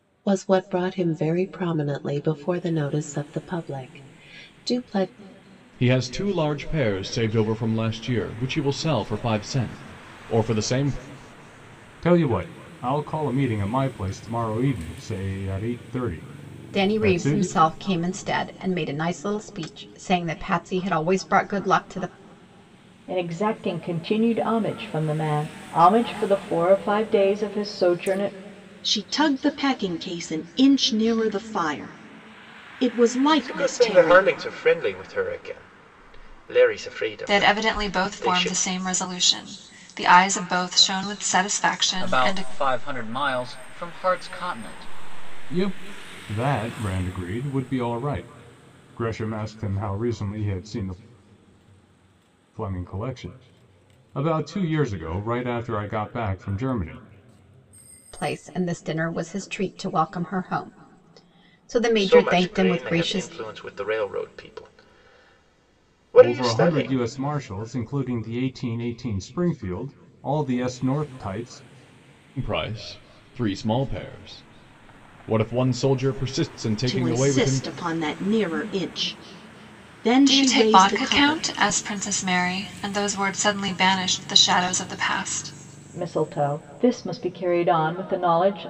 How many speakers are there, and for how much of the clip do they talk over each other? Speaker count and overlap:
9, about 9%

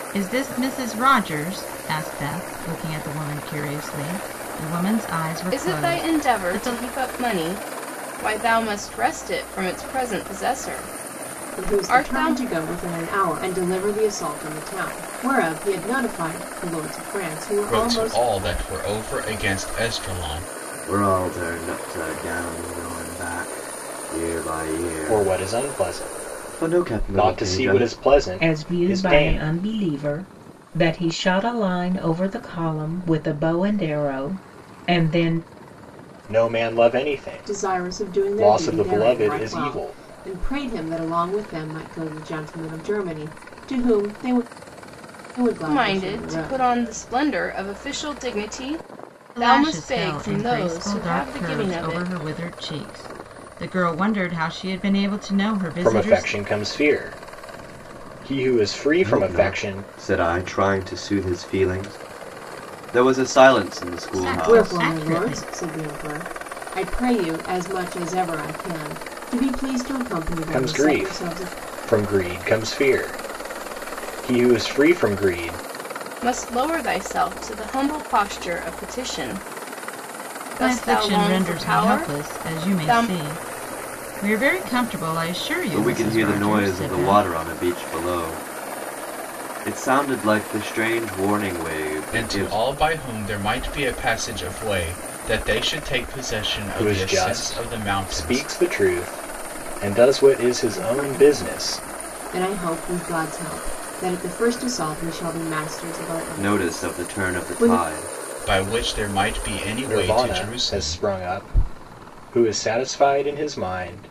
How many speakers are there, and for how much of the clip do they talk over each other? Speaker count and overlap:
7, about 24%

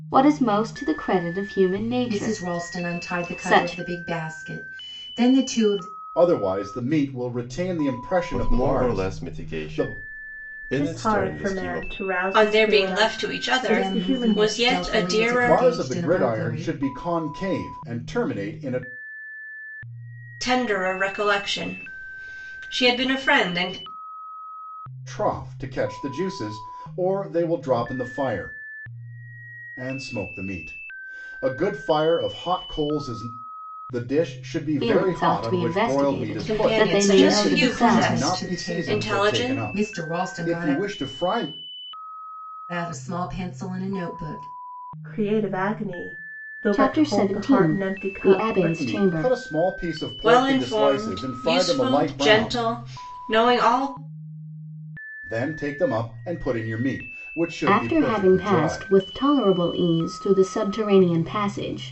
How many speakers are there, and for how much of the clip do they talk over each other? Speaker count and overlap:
6, about 35%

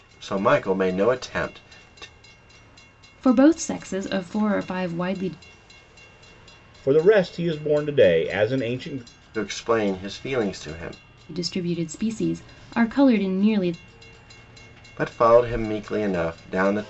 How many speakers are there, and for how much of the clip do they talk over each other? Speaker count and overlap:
3, no overlap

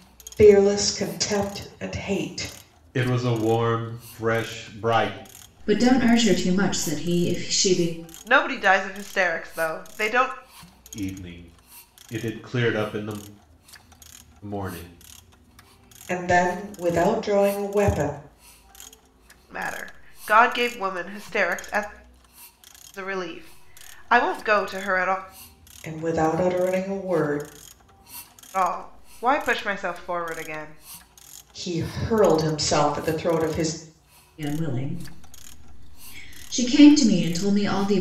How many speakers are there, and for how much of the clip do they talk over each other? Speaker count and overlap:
4, no overlap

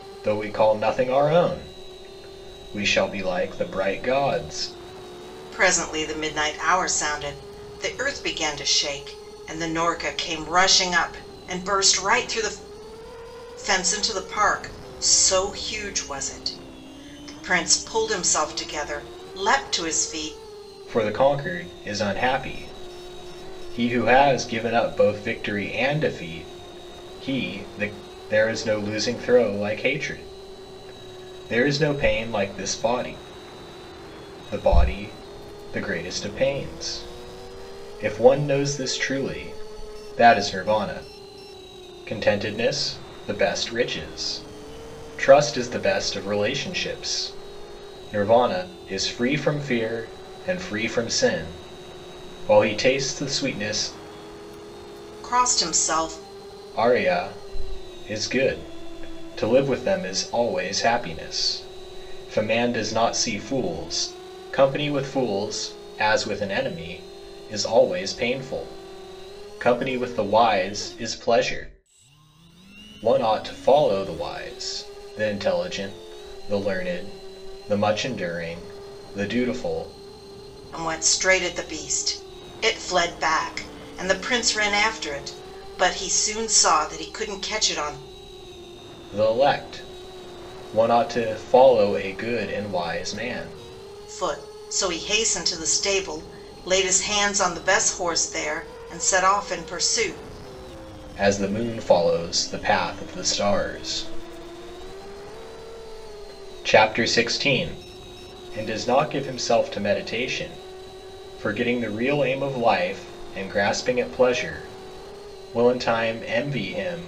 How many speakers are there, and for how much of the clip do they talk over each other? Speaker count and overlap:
2, no overlap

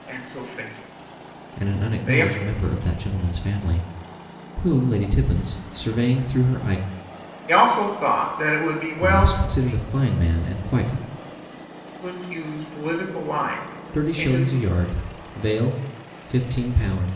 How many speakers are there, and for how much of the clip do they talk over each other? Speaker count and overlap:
2, about 11%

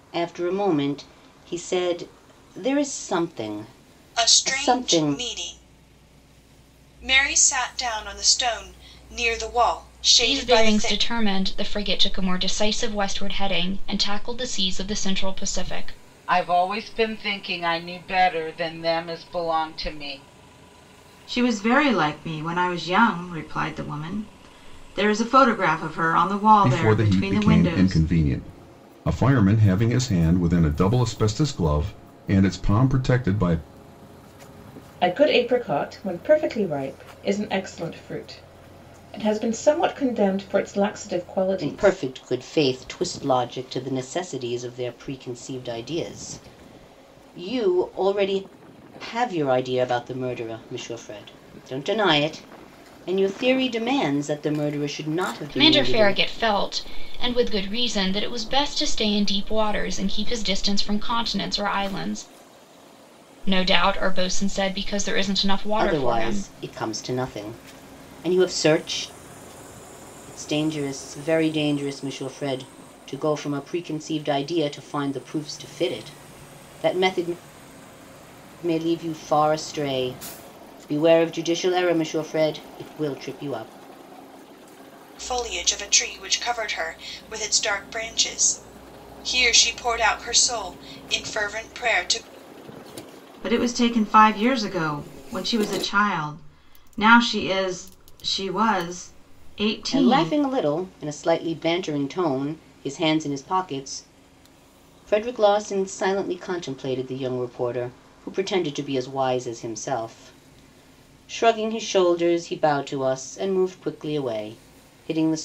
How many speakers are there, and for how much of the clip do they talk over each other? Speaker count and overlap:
7, about 5%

